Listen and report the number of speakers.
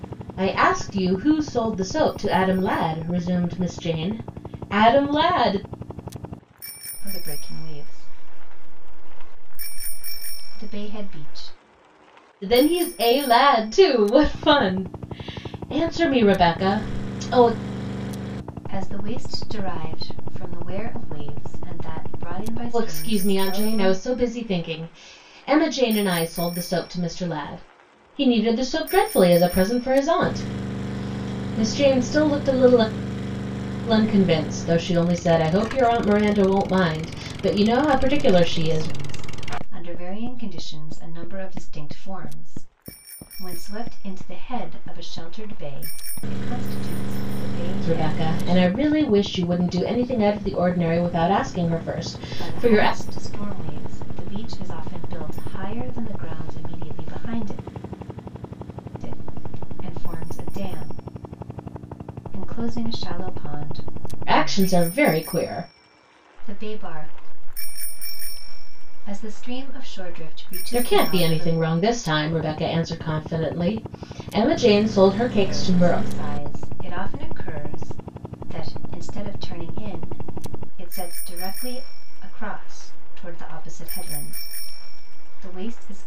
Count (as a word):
two